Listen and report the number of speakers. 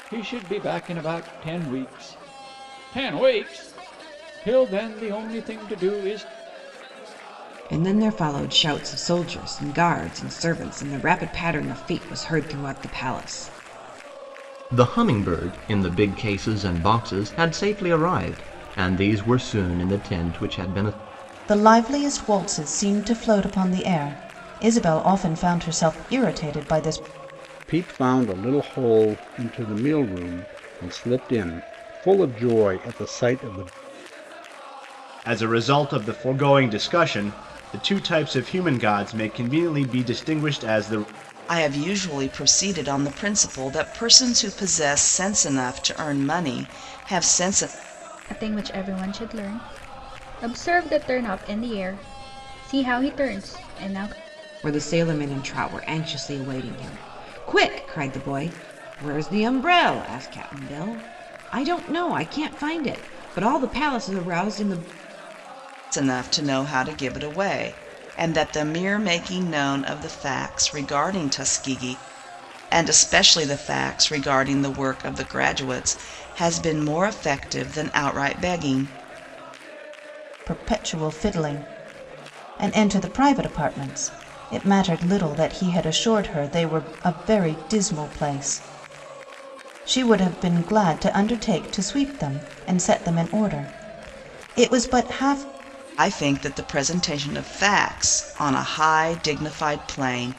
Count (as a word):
eight